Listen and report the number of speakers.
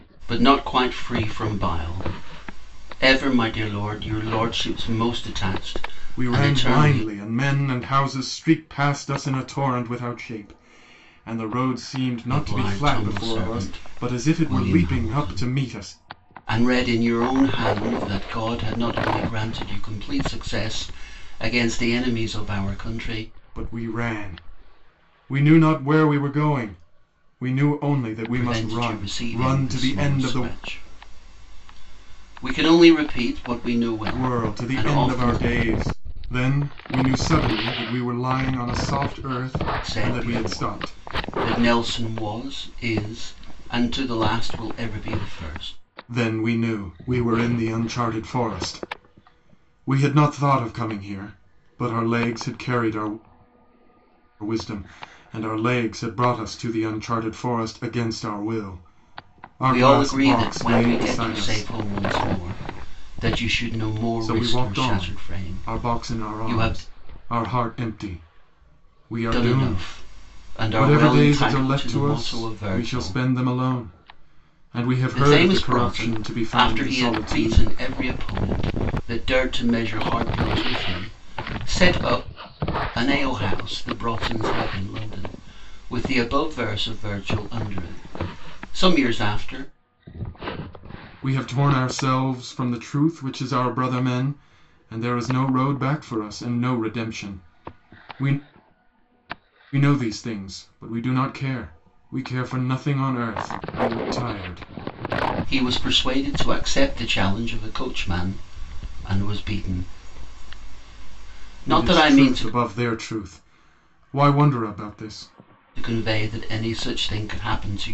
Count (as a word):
two